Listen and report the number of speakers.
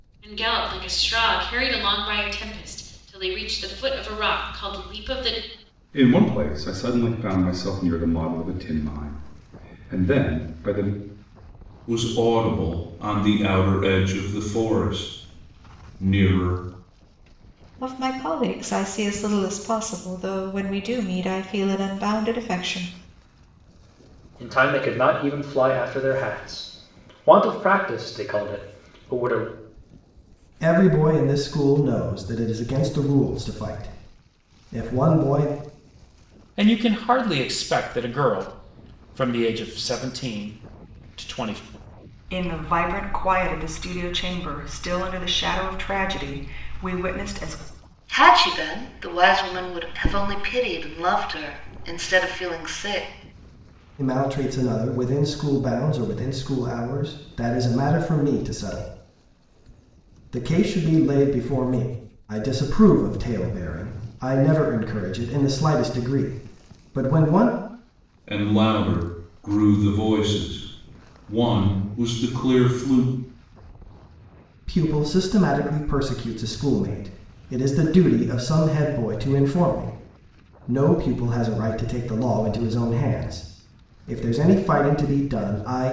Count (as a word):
nine